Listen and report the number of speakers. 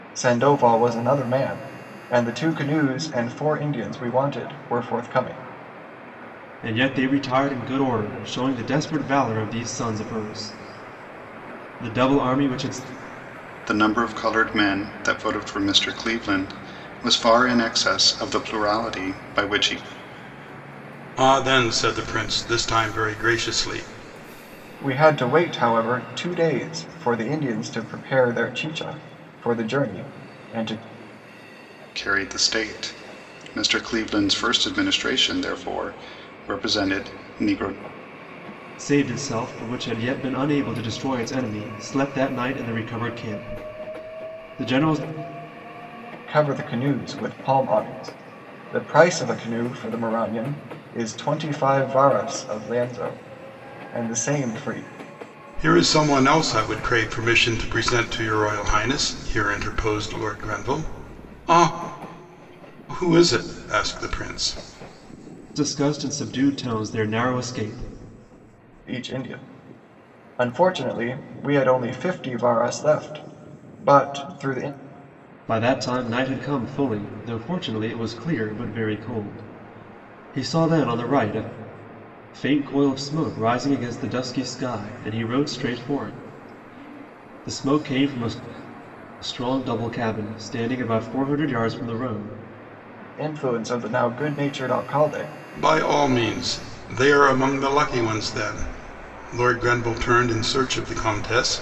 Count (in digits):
4